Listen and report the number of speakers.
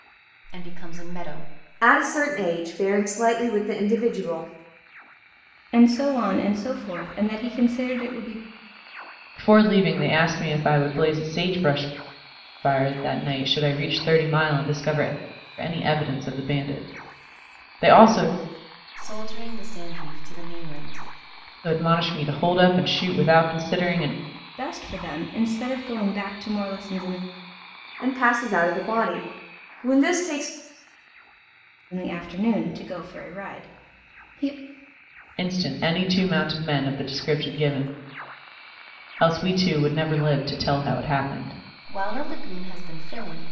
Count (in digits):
4